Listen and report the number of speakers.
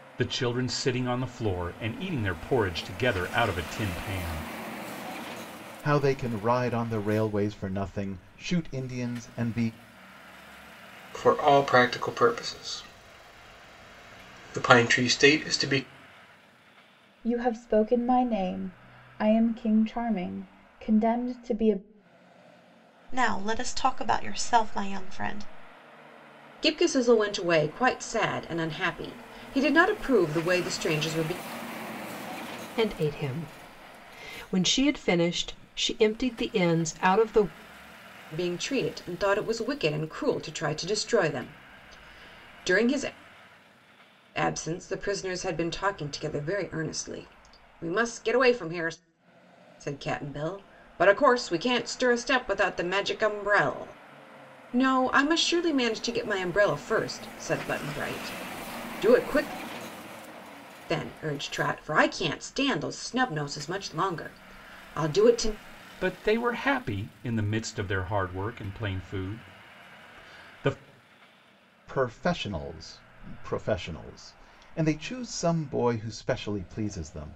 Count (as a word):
seven